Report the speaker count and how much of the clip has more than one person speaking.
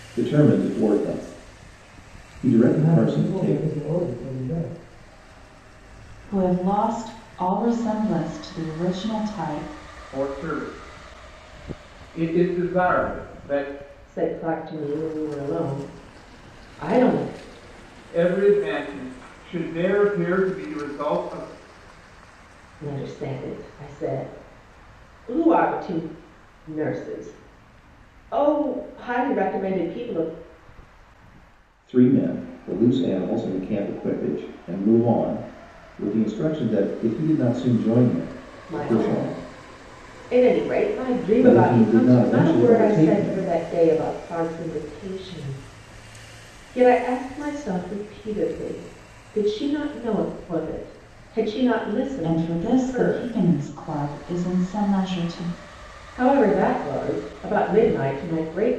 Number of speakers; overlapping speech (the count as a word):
five, about 9%